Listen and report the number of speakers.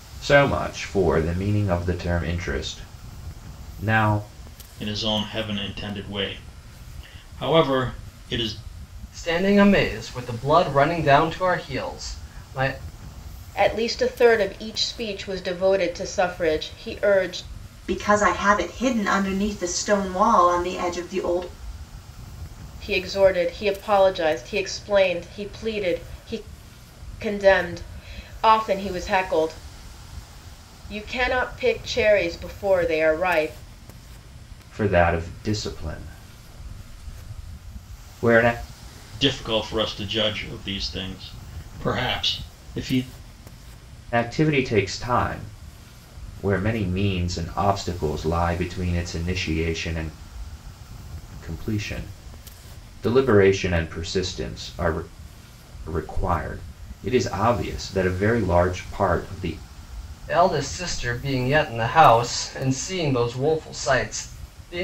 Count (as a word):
five